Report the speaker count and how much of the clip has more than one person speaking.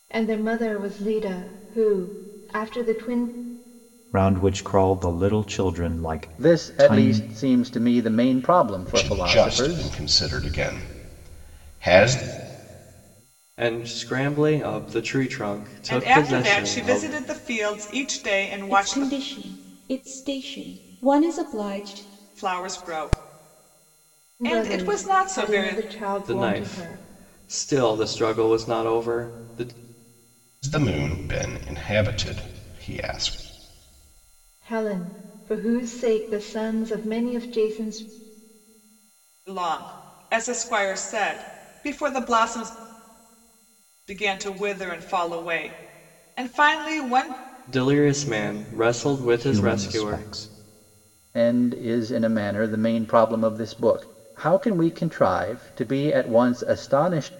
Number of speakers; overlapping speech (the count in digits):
7, about 12%